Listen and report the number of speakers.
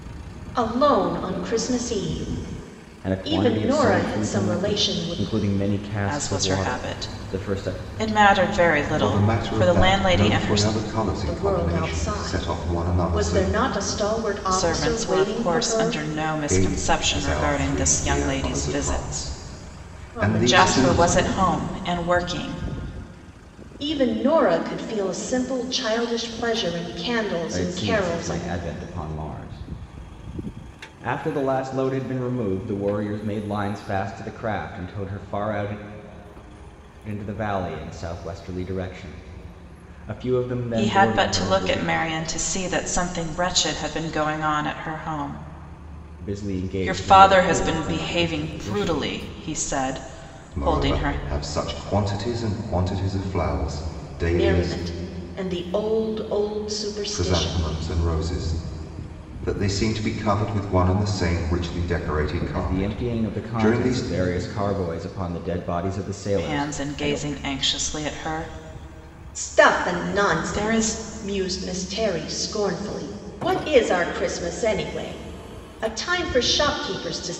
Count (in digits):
4